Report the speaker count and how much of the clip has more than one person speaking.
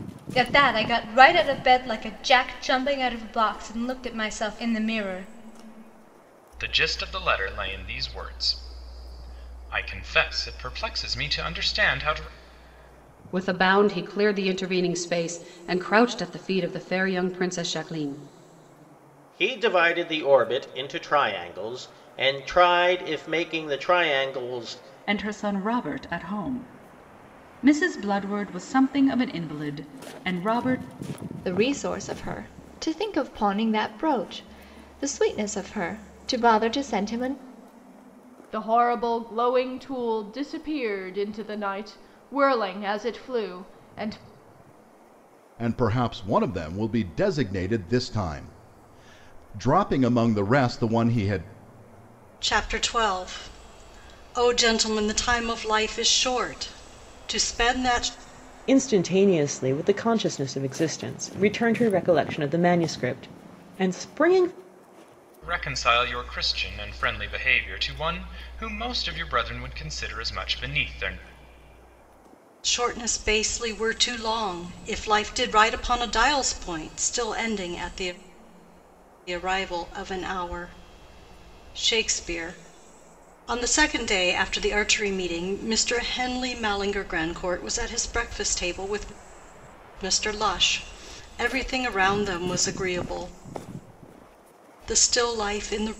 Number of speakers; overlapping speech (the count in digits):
10, no overlap